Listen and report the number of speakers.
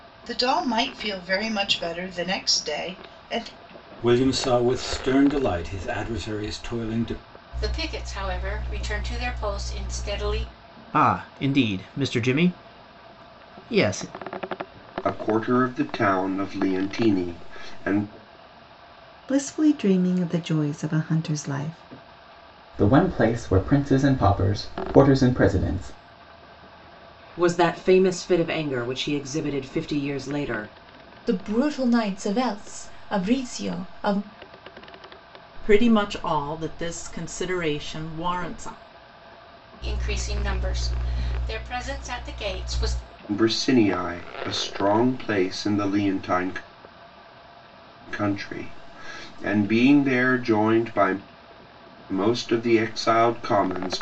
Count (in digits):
10